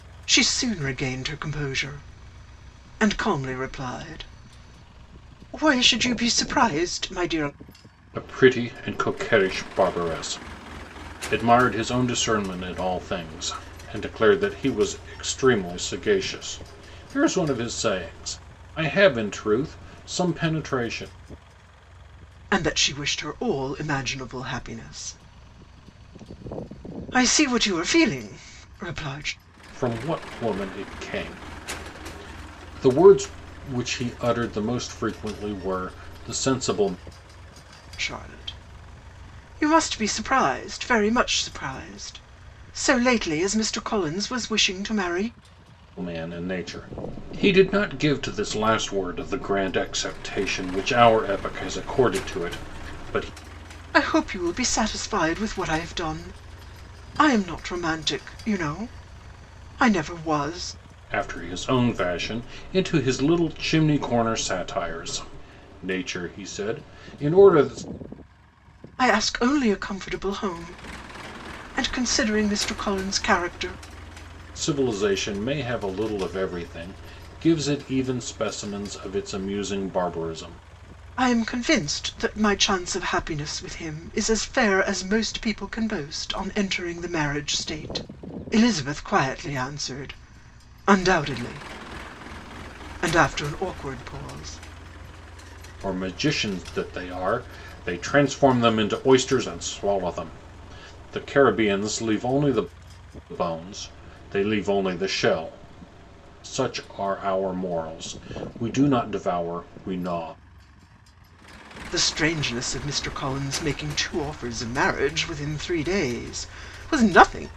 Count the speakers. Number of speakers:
two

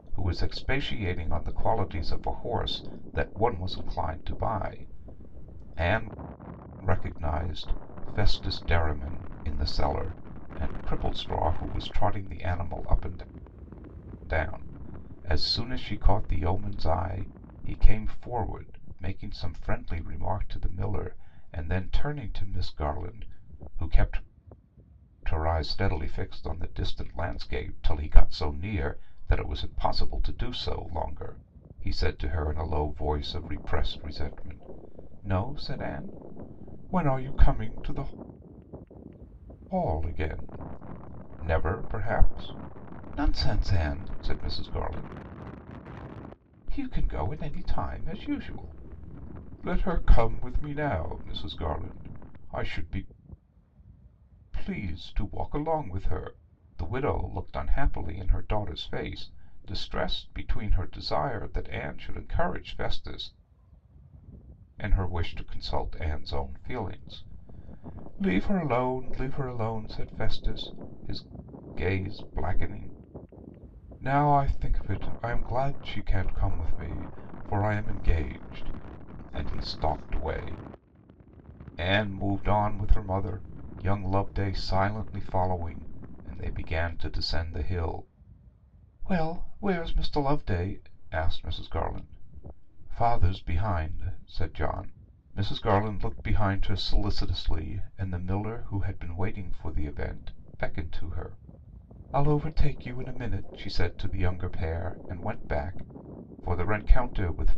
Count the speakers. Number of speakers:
one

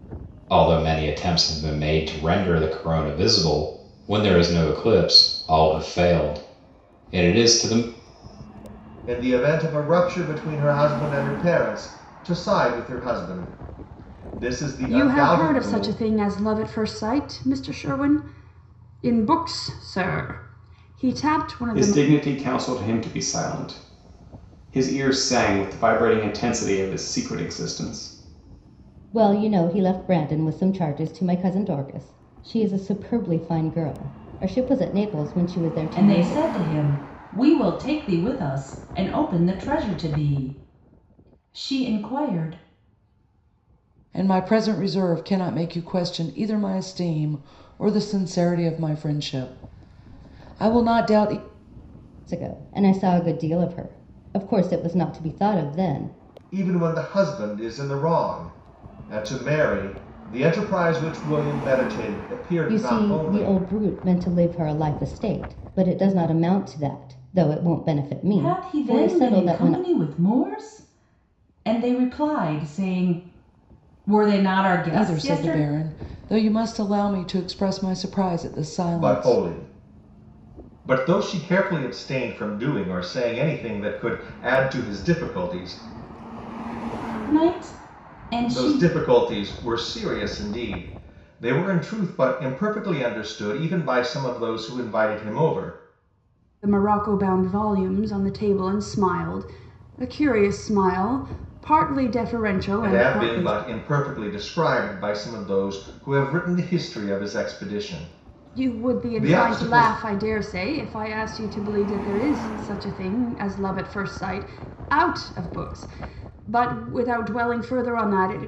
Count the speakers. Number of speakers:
seven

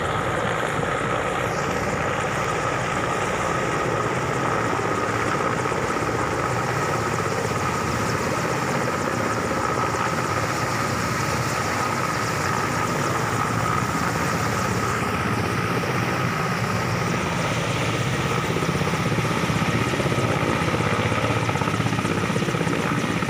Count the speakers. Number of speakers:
zero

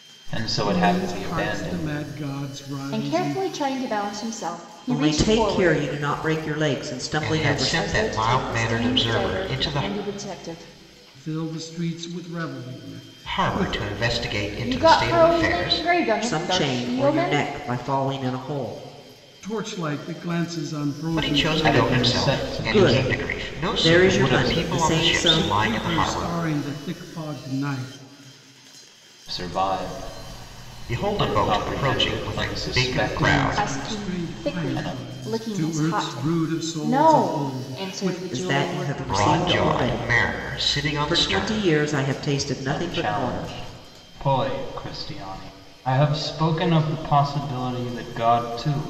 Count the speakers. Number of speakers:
five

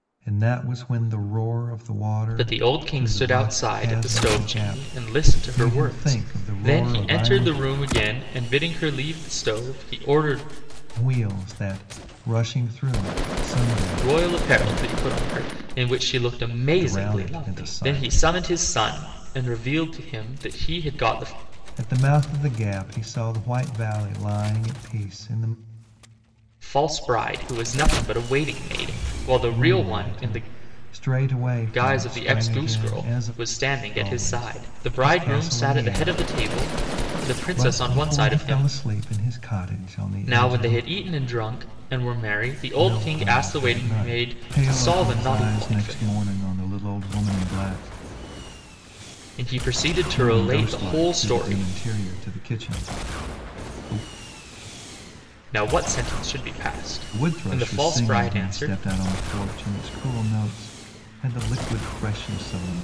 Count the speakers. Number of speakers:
two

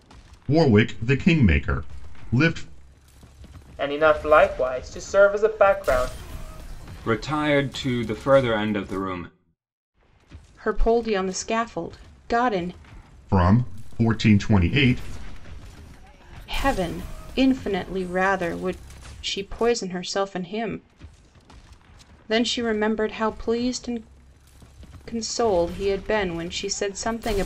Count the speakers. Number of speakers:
four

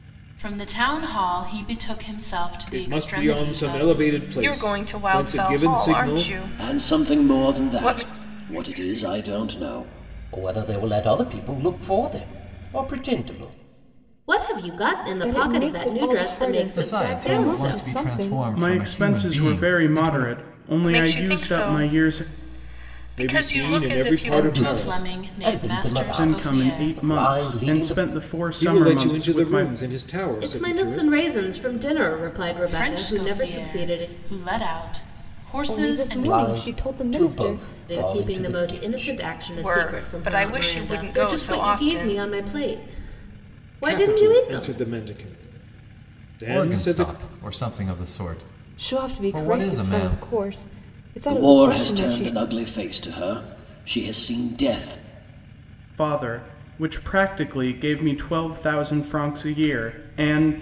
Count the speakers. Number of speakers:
nine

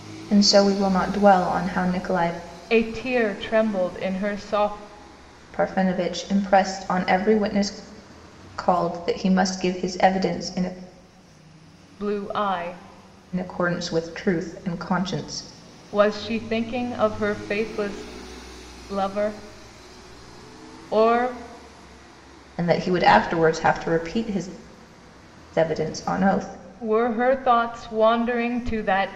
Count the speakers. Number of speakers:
two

